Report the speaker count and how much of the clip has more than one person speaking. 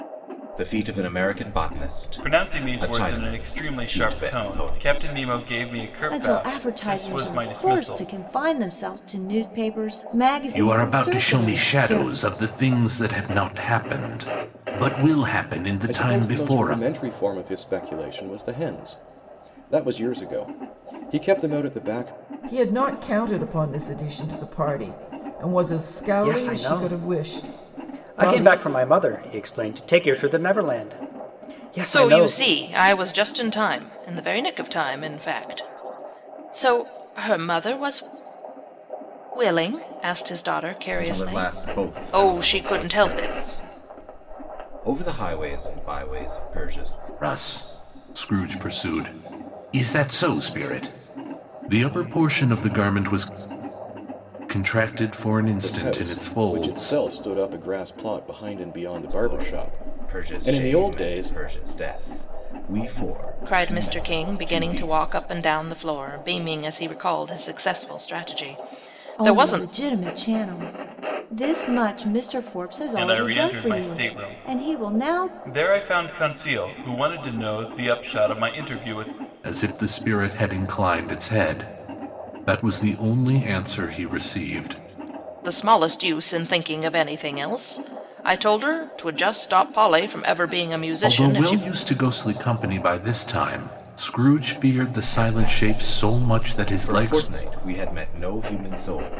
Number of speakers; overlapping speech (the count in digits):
8, about 25%